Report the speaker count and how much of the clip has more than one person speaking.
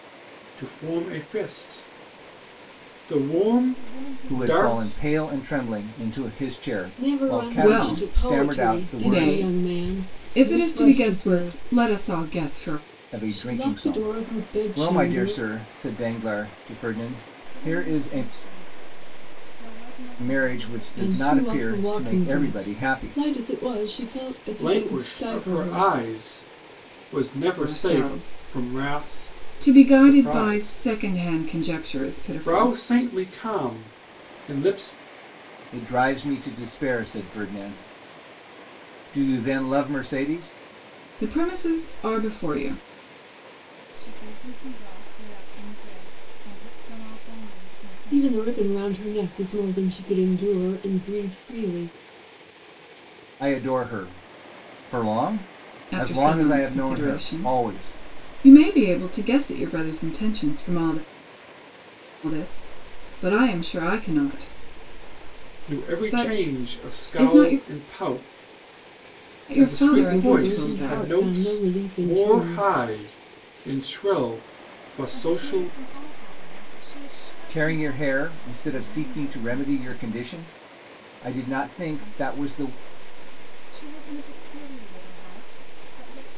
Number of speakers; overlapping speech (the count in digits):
5, about 36%